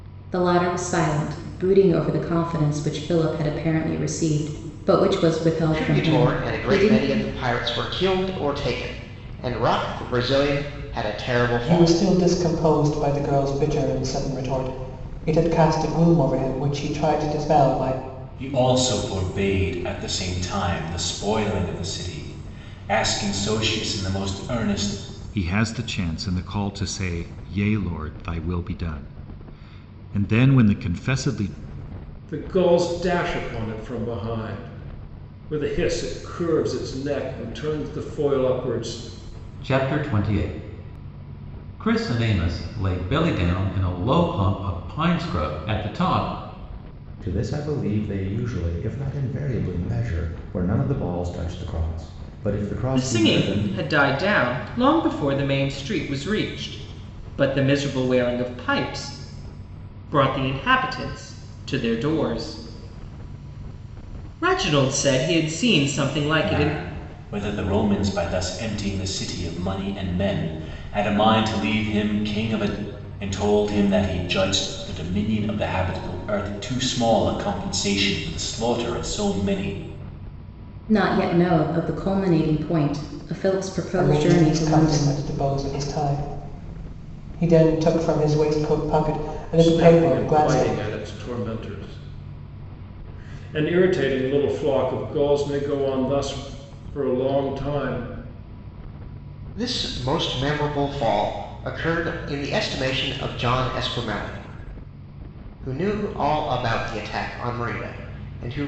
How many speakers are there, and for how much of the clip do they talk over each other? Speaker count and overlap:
9, about 5%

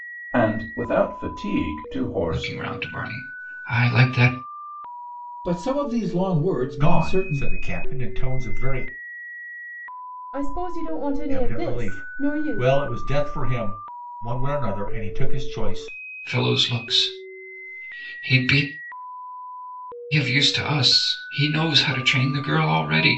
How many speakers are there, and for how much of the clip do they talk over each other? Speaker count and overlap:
5, about 10%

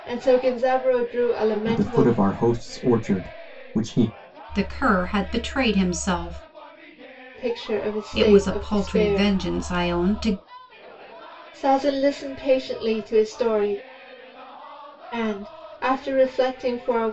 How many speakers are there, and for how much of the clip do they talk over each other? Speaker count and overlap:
3, about 10%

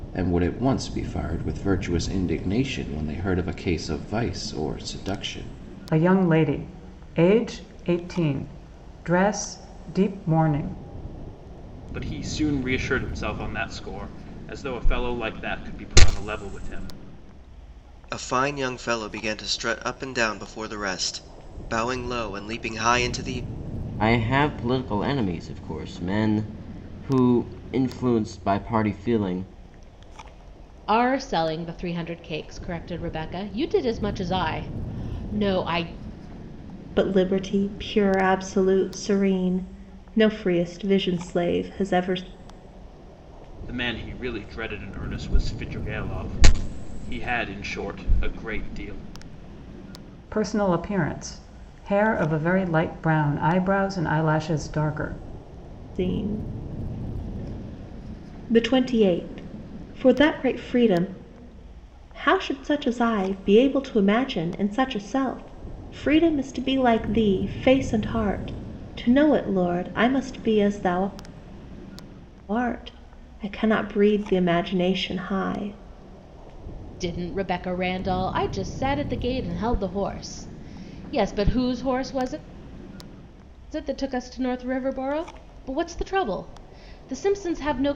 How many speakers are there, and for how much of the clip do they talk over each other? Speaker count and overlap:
7, no overlap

